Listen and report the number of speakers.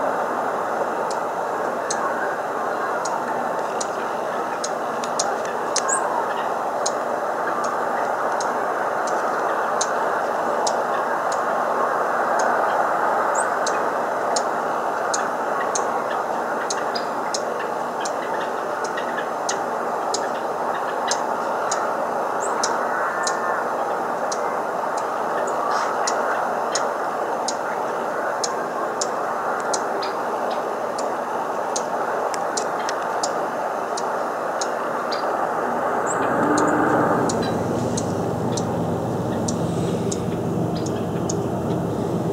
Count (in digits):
0